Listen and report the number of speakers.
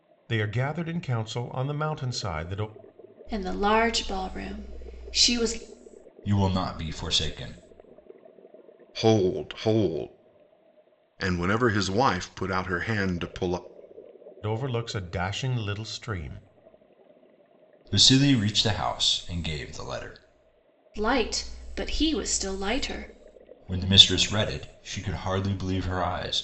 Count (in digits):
4